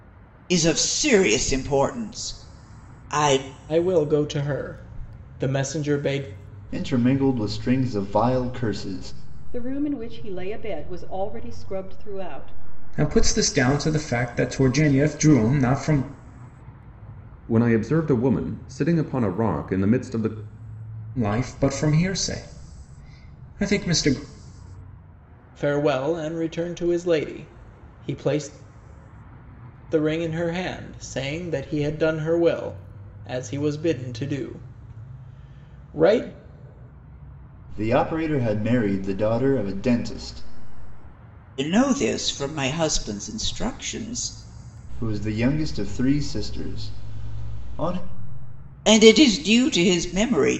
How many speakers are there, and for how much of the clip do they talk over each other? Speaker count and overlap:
six, no overlap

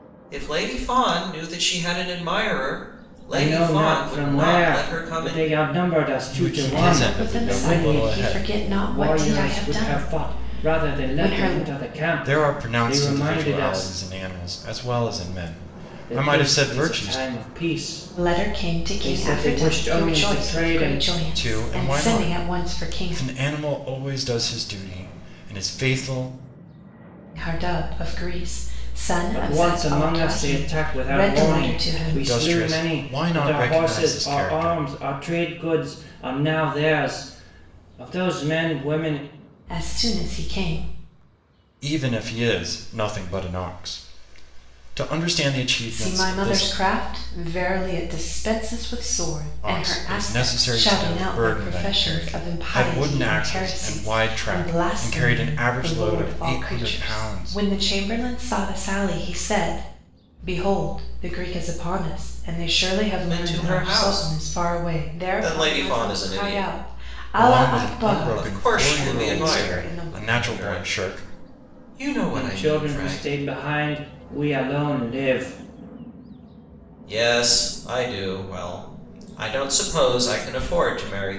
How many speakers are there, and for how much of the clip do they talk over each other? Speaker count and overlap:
four, about 46%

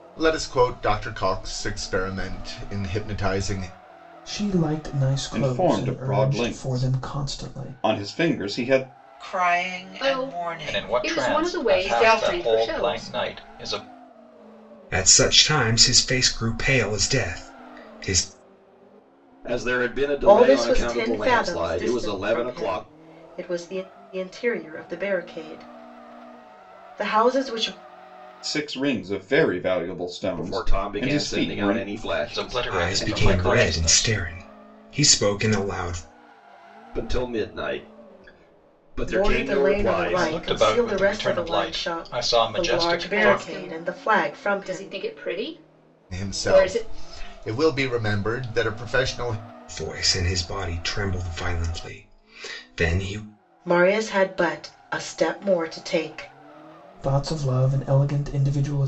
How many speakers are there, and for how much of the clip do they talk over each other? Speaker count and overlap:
nine, about 31%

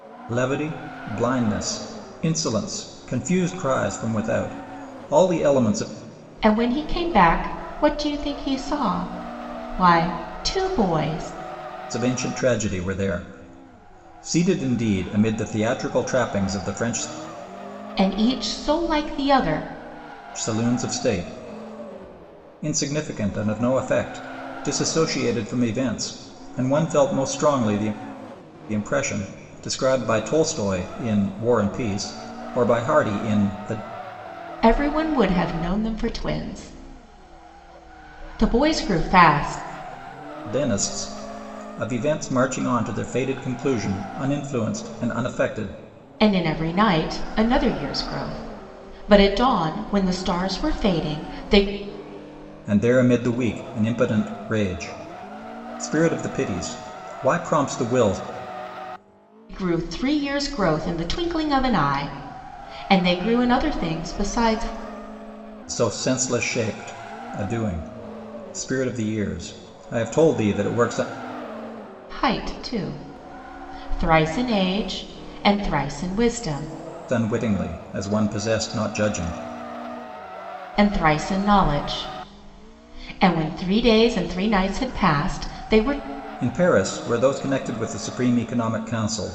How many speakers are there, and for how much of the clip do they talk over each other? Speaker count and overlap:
two, no overlap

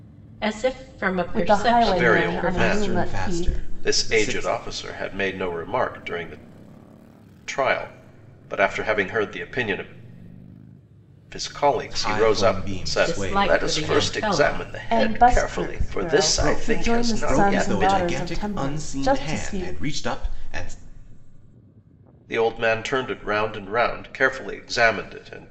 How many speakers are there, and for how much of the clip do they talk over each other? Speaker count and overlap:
four, about 43%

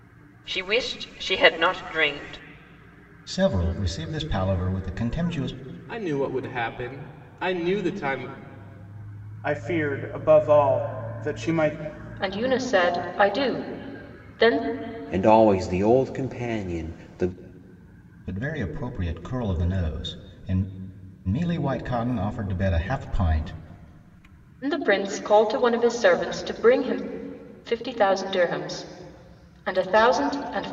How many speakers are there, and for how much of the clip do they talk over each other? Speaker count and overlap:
six, no overlap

